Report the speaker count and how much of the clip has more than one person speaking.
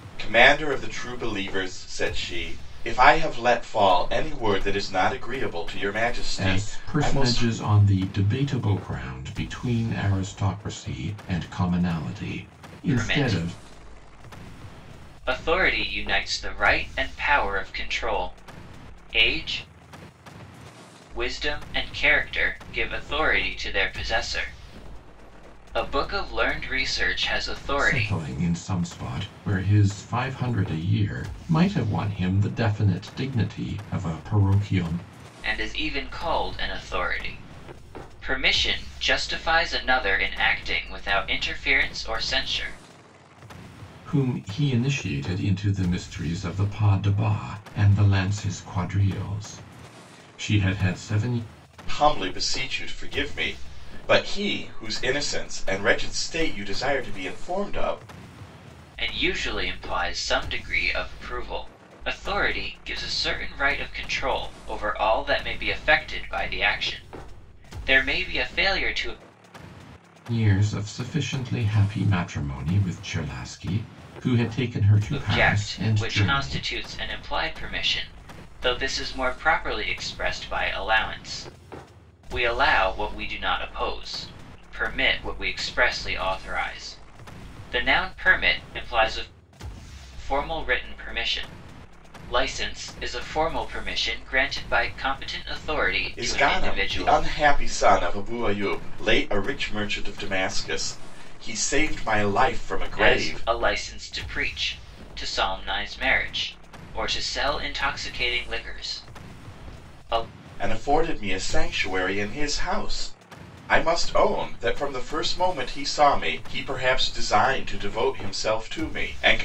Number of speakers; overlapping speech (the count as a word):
three, about 4%